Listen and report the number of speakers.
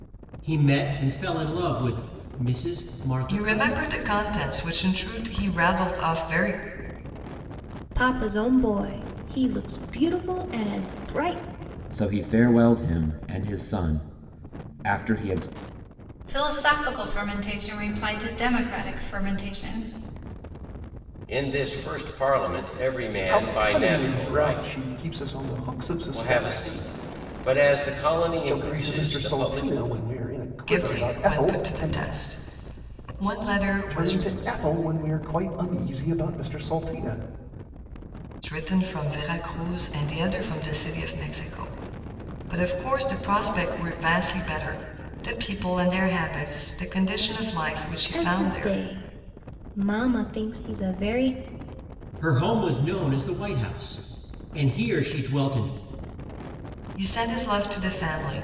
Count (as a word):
seven